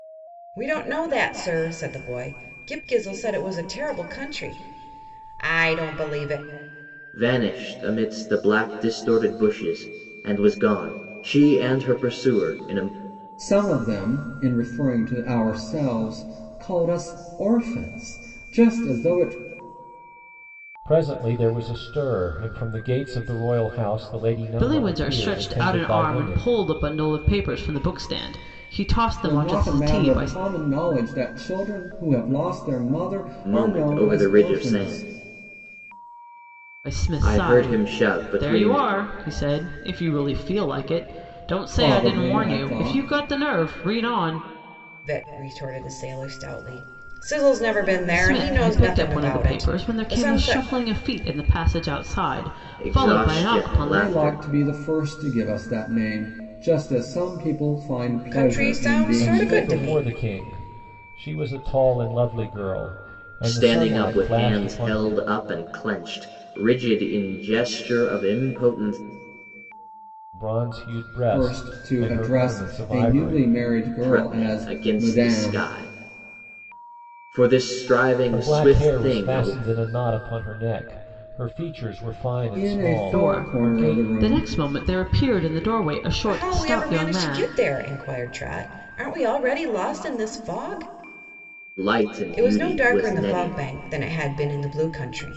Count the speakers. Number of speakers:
5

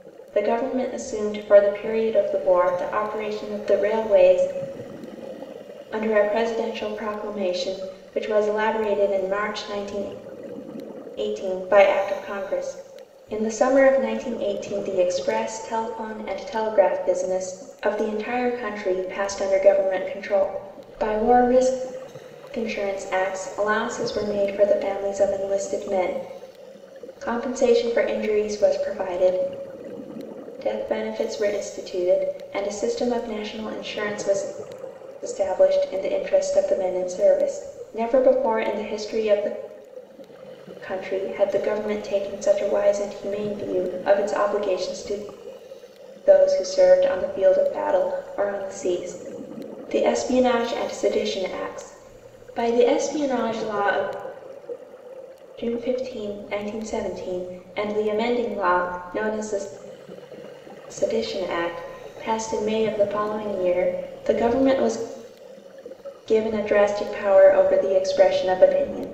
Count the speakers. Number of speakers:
1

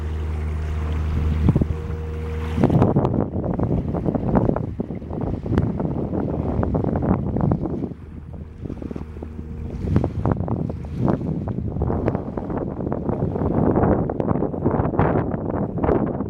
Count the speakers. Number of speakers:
0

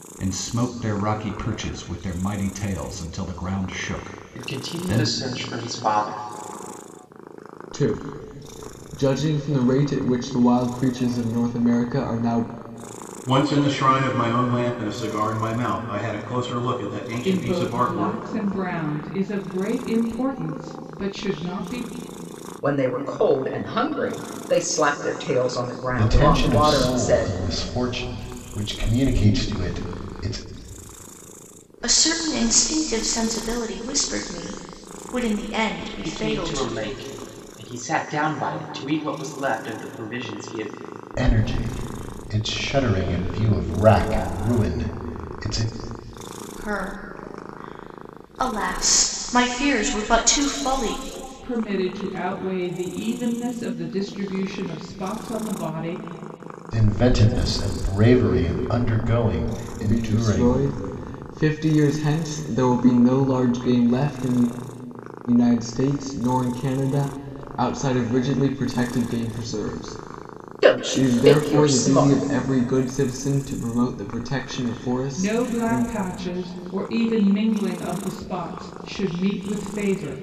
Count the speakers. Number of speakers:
8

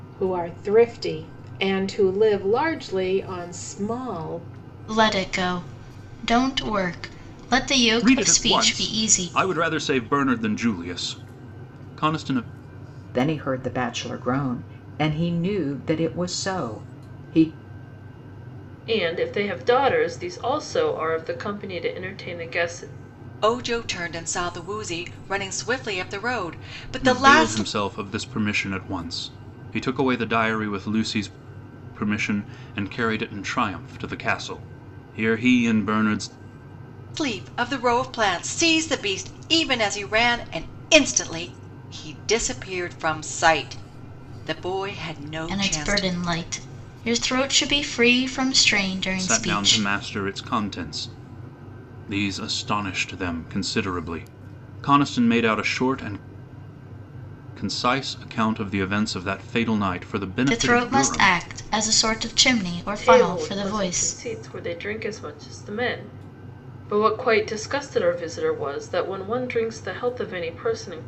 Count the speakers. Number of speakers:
6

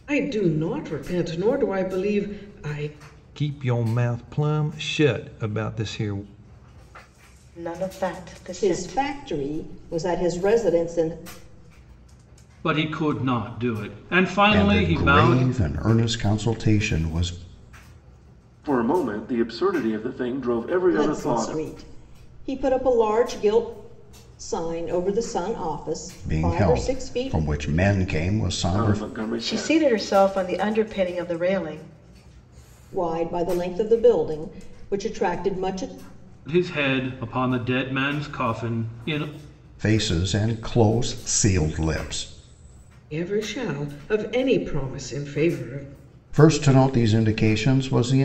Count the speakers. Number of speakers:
7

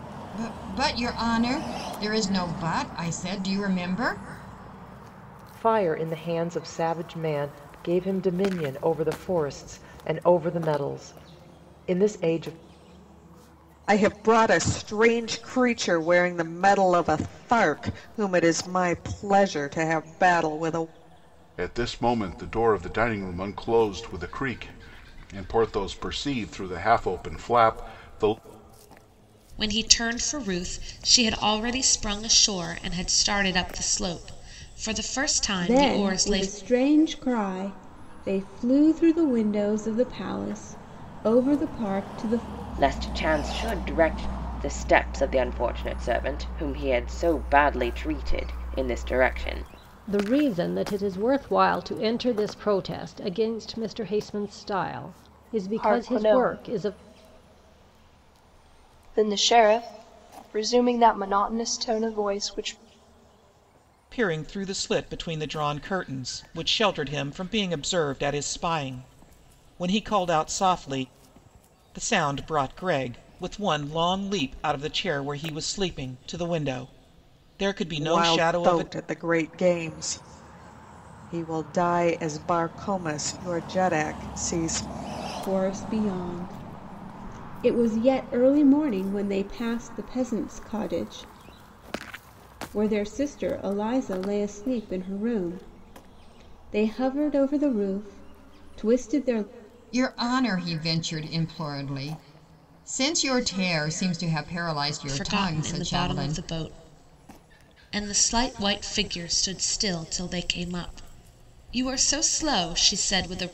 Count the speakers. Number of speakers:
10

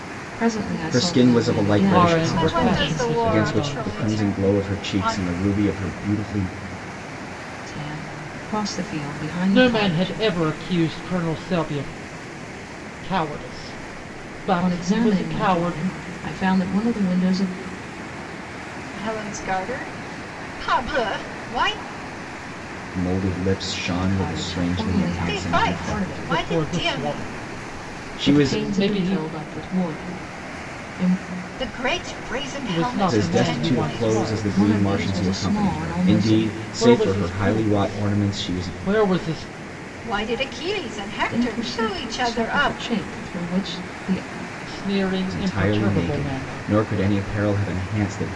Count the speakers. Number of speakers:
4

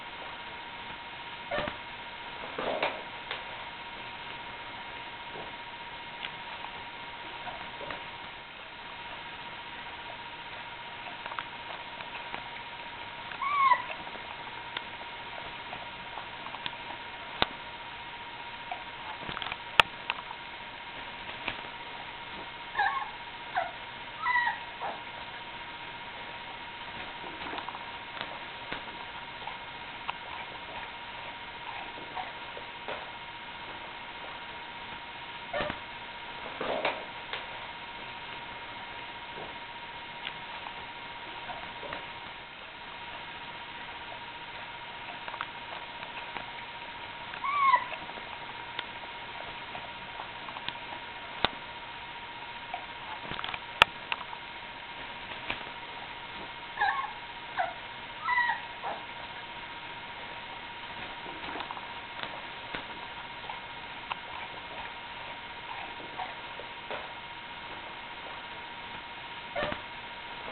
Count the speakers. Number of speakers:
0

